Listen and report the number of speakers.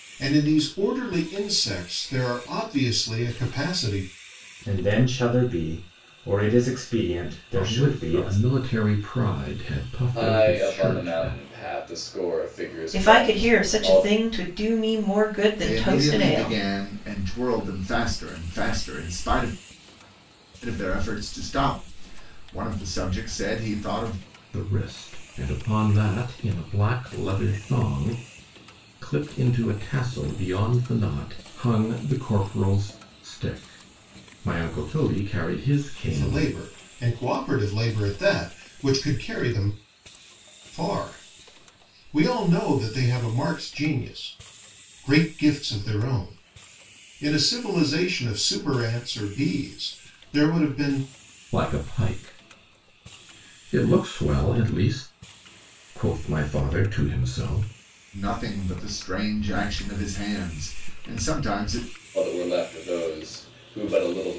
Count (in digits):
6